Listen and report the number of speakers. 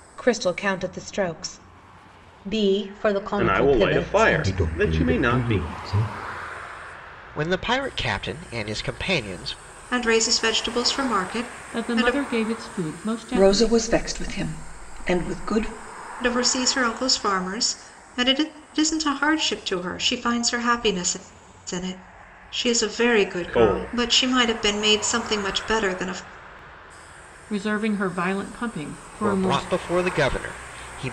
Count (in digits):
8